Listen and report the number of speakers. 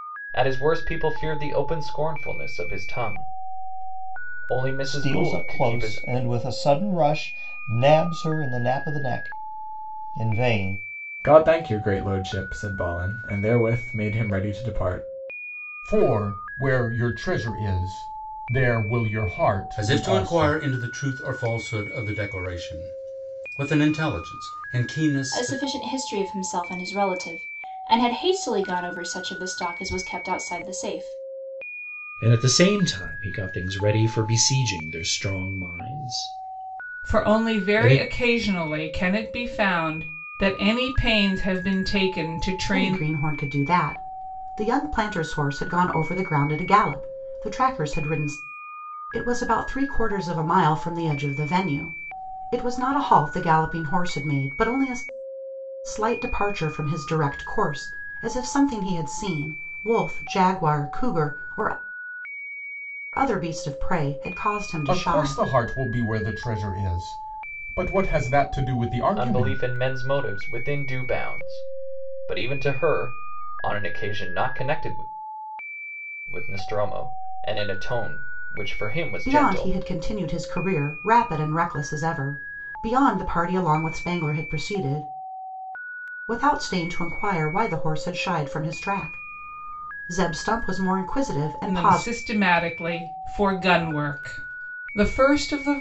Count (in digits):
9